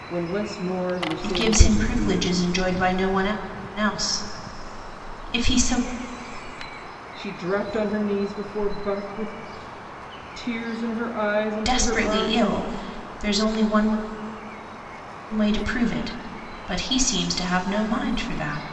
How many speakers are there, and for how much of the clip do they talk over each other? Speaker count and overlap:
two, about 12%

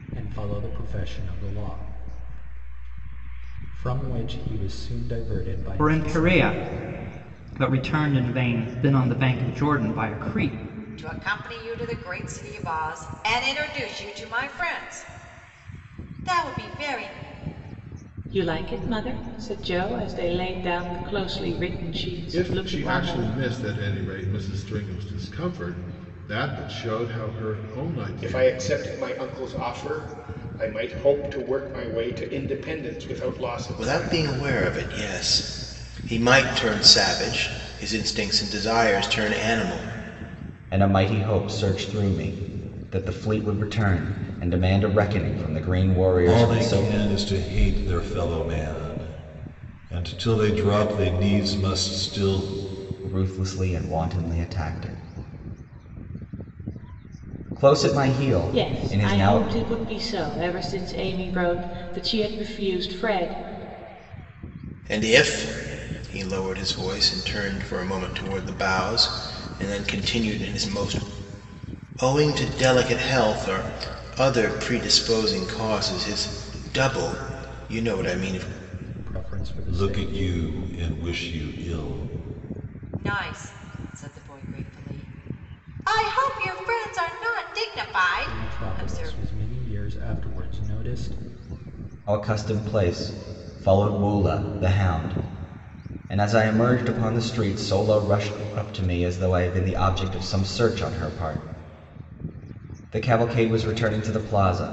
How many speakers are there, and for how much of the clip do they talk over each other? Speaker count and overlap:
nine, about 6%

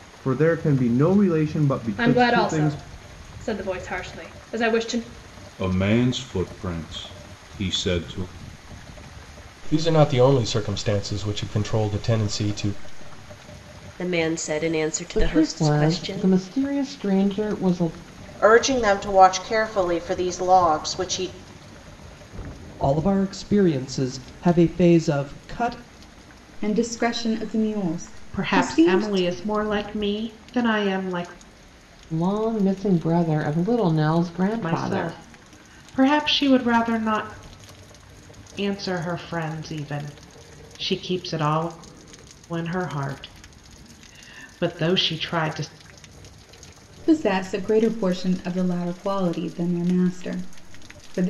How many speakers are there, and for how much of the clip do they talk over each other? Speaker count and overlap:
ten, about 7%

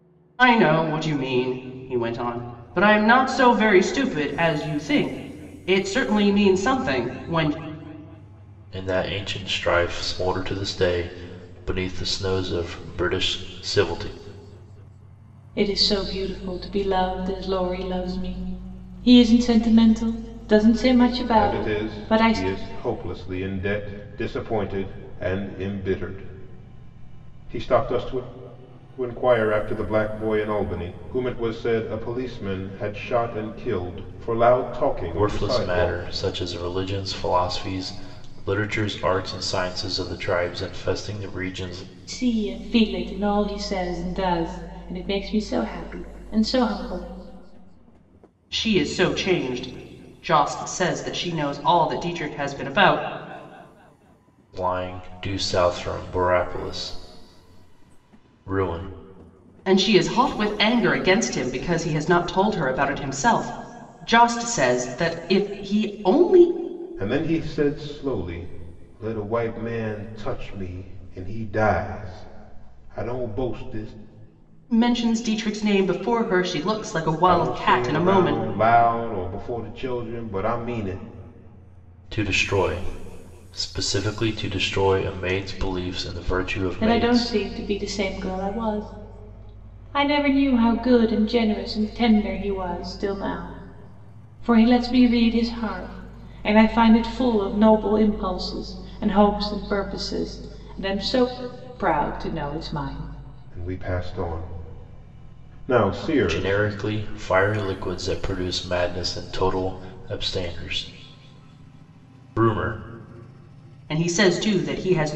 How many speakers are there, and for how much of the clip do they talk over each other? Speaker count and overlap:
four, about 4%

